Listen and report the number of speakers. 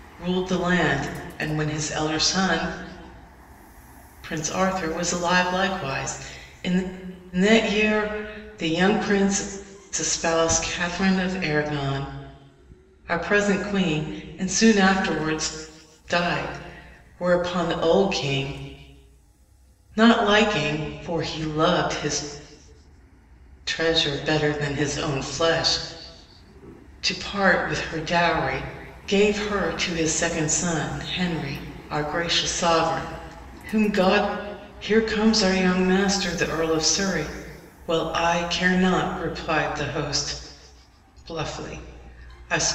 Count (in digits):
1